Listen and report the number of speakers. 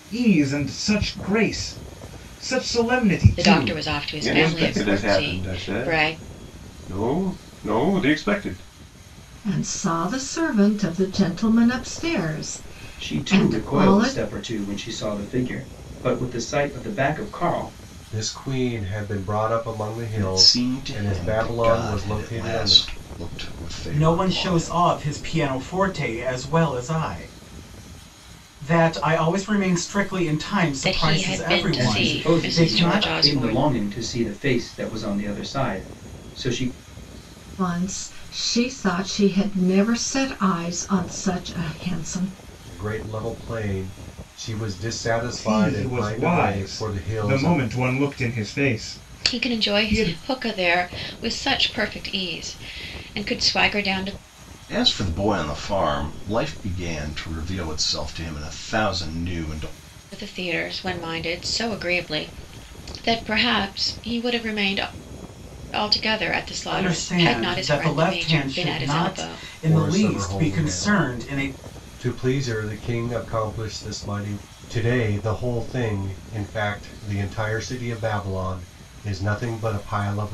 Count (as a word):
eight